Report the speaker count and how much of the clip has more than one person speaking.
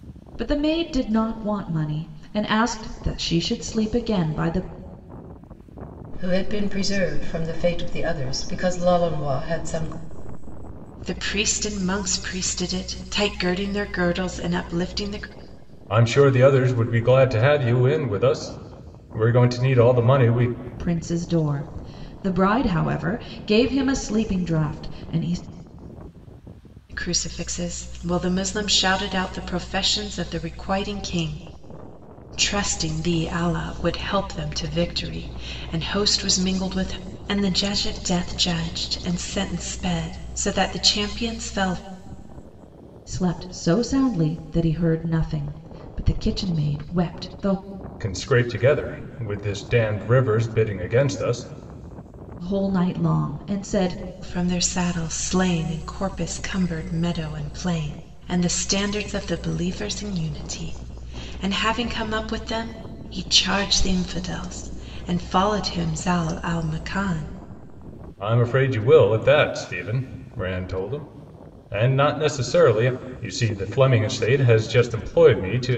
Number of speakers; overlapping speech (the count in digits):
4, no overlap